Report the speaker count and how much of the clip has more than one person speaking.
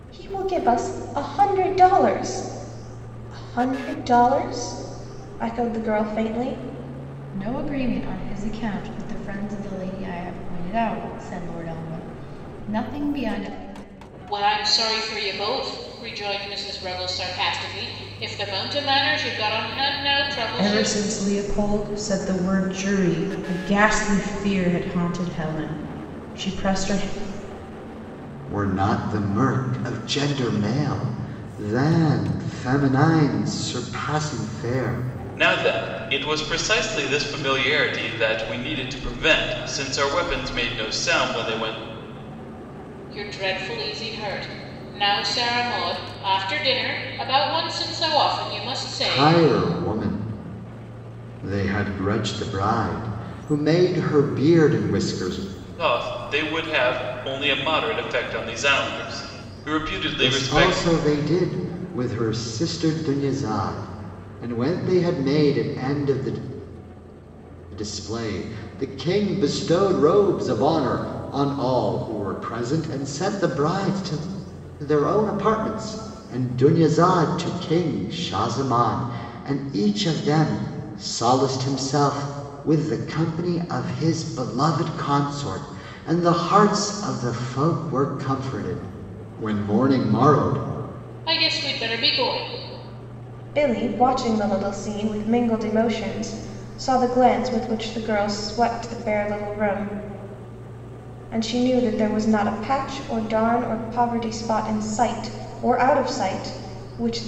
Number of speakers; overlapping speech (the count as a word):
six, about 1%